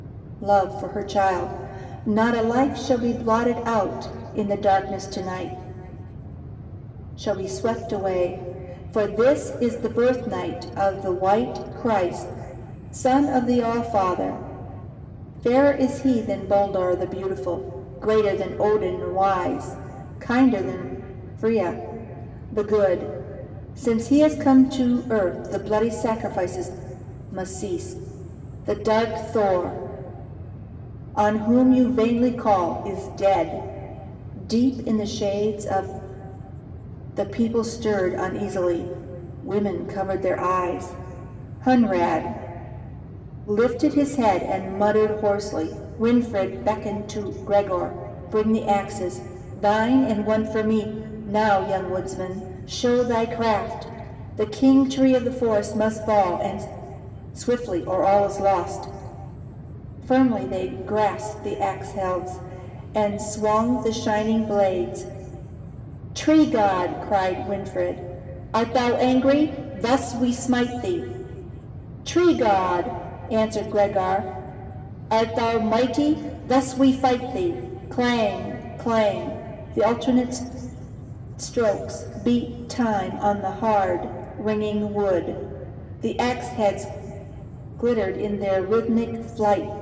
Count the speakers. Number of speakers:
one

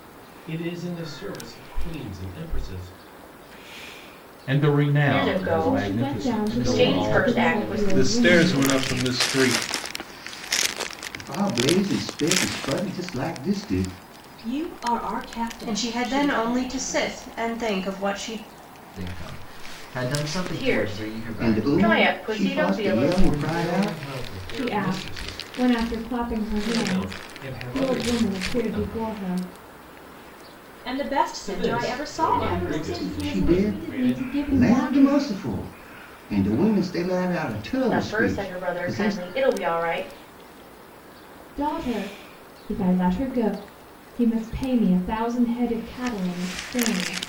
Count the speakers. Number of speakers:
nine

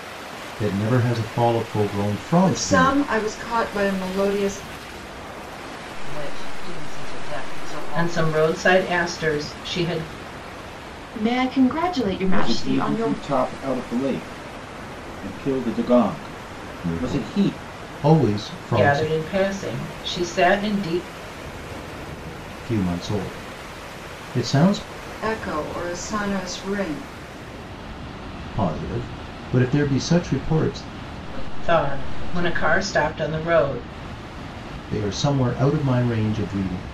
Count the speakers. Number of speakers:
six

